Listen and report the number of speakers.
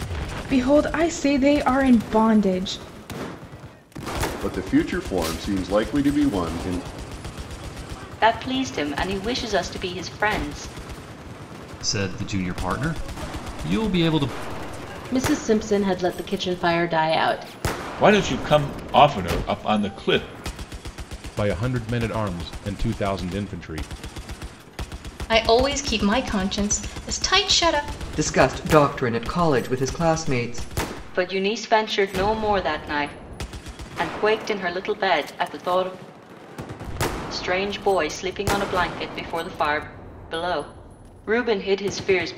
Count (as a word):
nine